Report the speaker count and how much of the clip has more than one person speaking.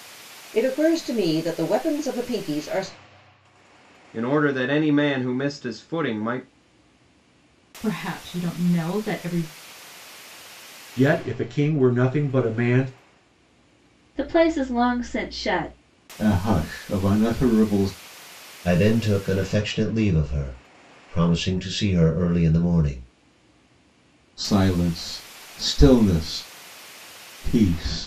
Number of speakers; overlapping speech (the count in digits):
7, no overlap